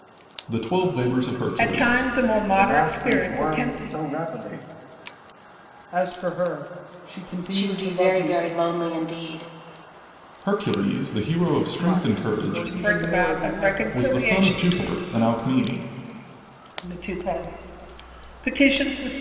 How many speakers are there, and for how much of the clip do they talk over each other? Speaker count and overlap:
five, about 33%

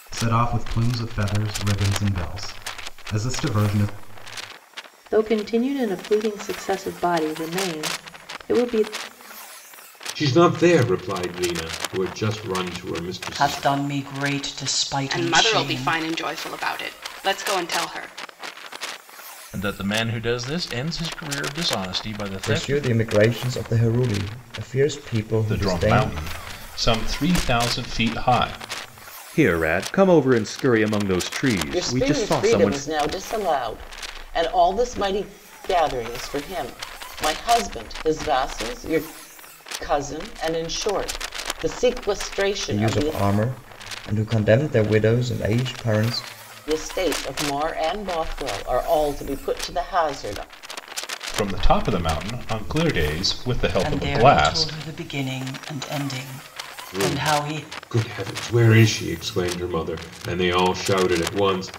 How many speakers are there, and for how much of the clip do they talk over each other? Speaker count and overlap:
ten, about 10%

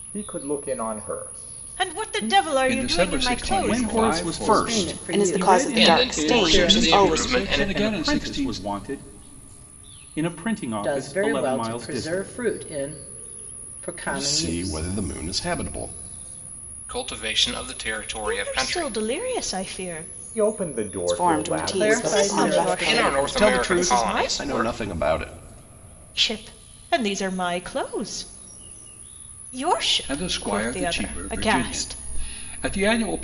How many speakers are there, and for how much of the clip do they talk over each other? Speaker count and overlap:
eight, about 47%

